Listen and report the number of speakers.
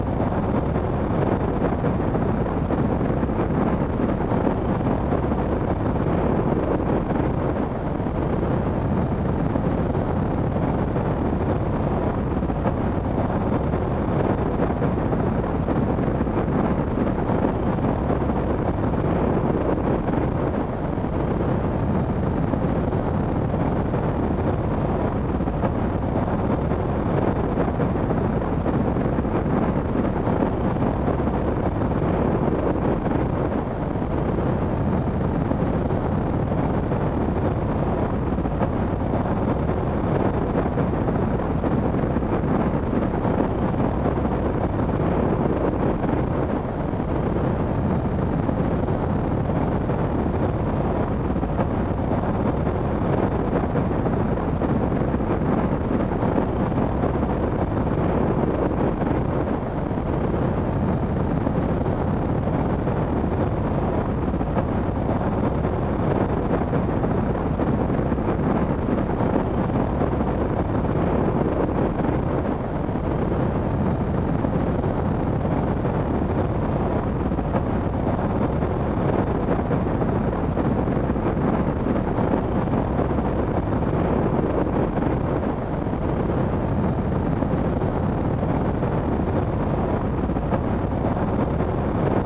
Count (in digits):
0